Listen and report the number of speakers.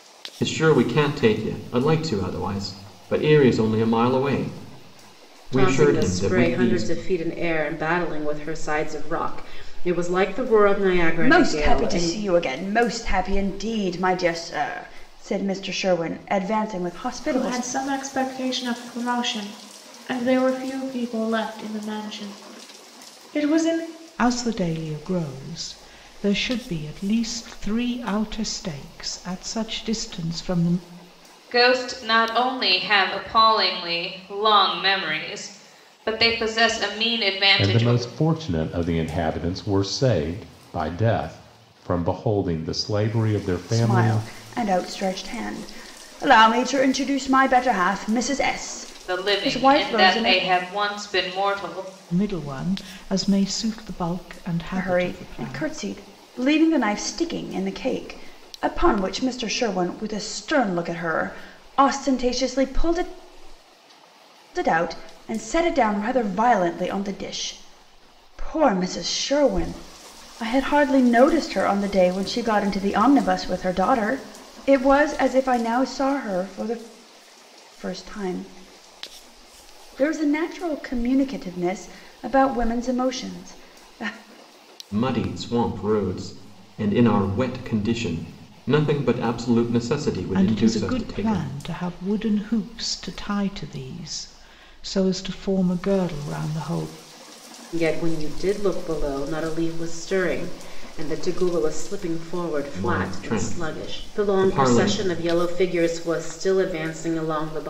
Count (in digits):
7